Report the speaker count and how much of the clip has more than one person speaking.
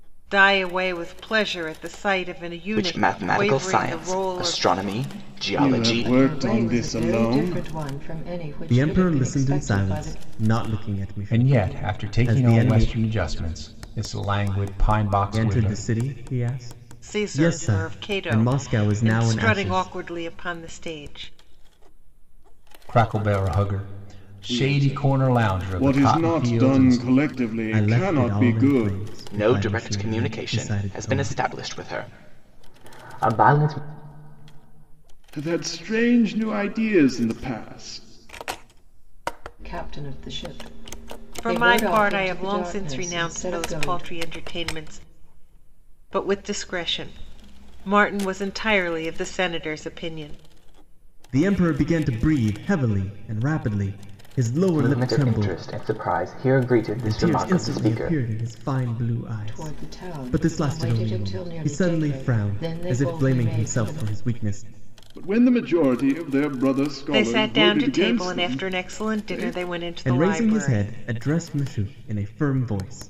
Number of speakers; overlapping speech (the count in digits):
6, about 40%